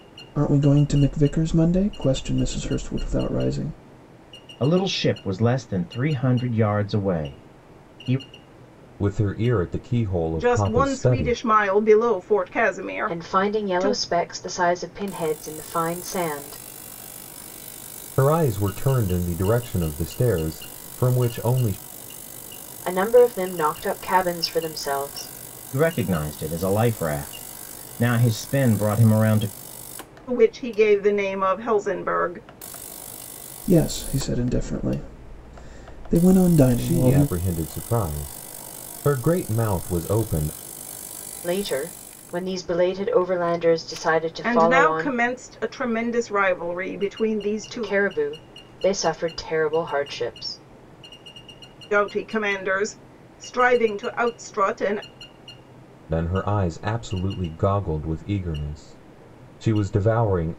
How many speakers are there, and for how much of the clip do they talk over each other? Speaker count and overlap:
5, about 6%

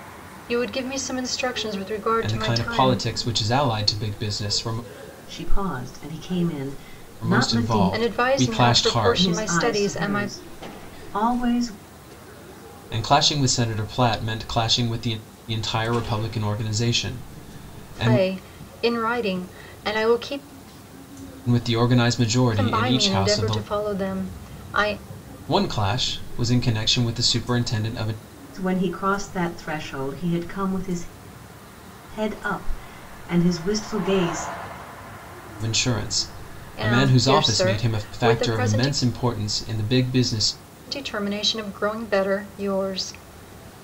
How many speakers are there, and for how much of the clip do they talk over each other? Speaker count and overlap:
3, about 17%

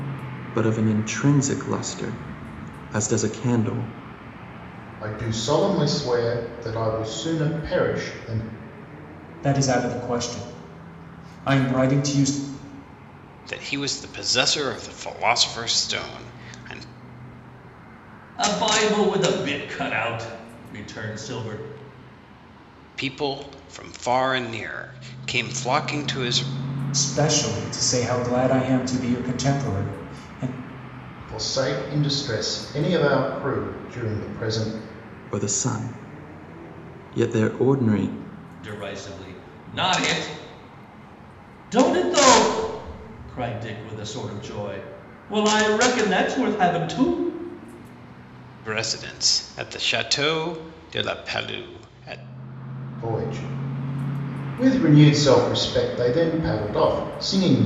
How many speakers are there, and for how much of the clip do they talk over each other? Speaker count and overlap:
5, no overlap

